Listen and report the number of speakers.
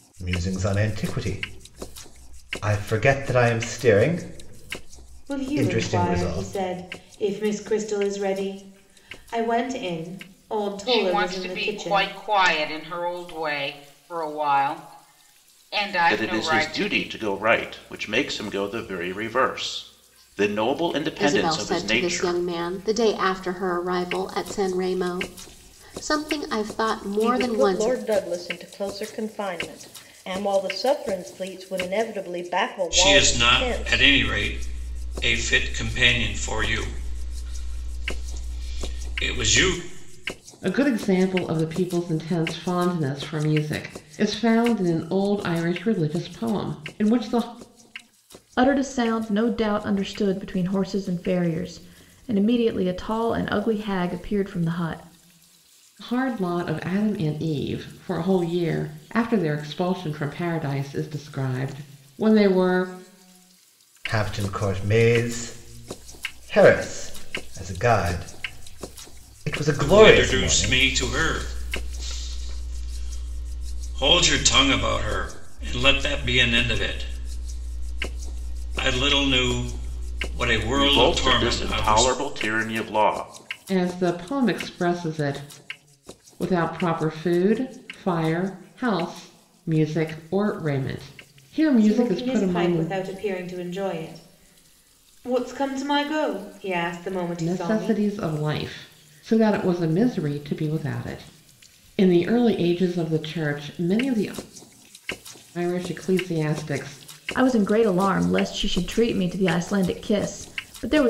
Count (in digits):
9